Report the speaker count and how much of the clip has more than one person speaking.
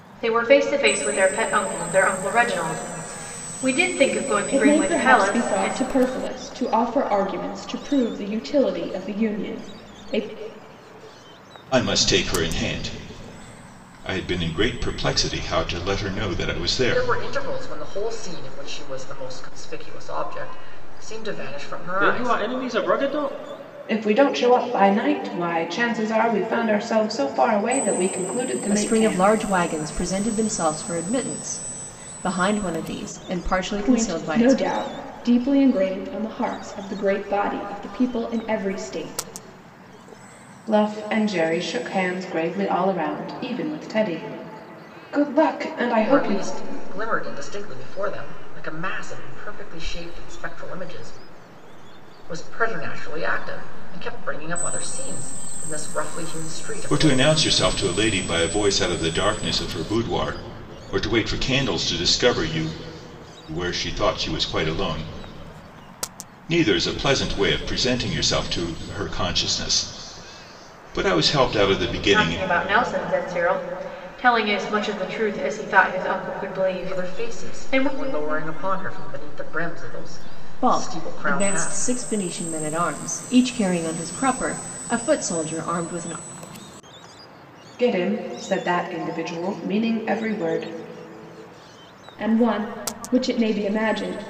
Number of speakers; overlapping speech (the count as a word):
seven, about 8%